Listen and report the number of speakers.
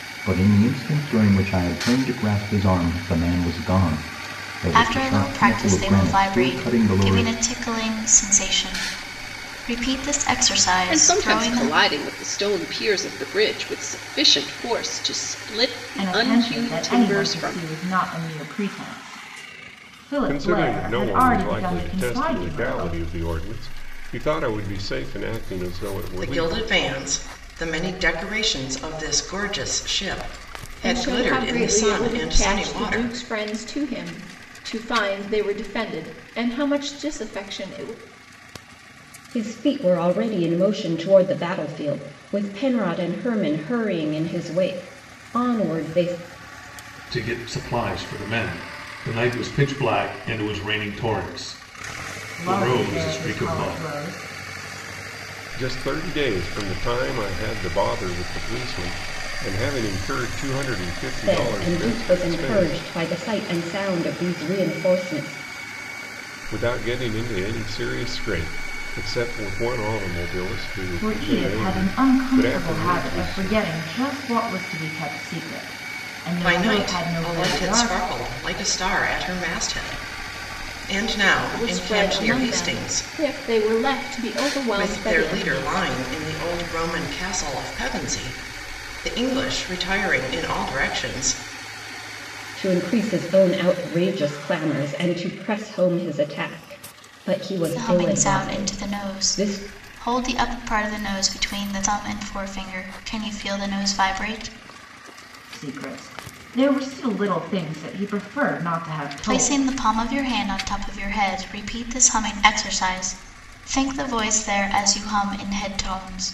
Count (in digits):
9